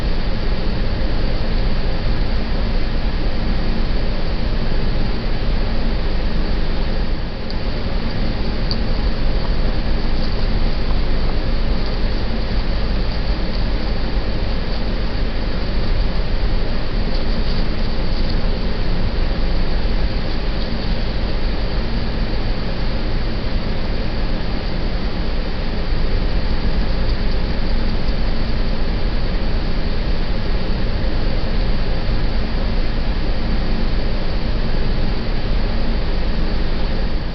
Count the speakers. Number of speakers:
zero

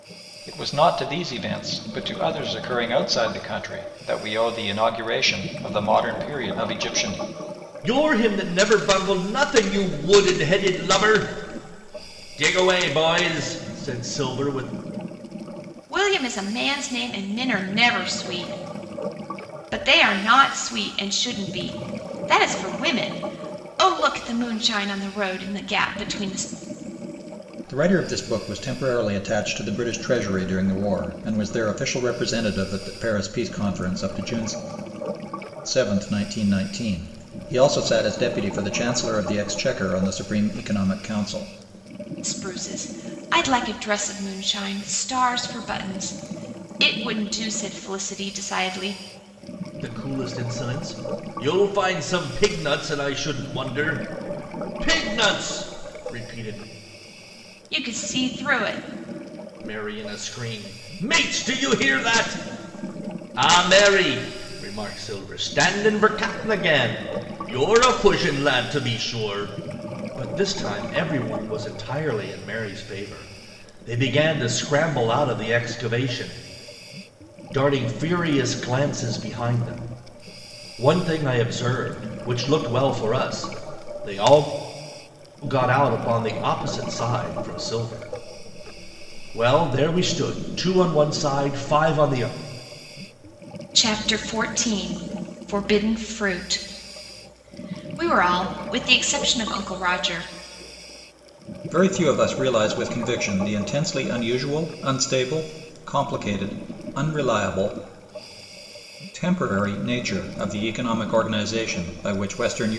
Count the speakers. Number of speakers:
three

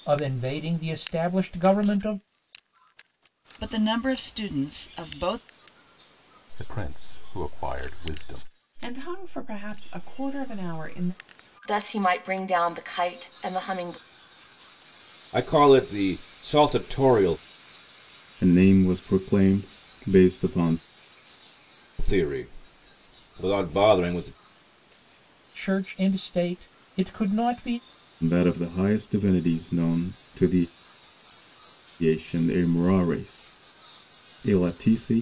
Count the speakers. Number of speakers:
seven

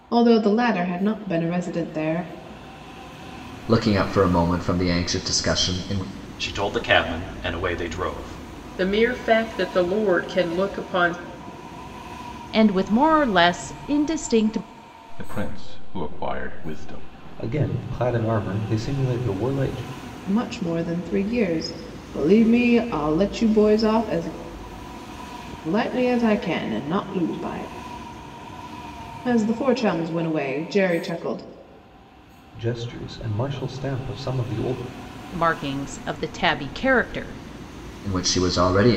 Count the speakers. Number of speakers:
seven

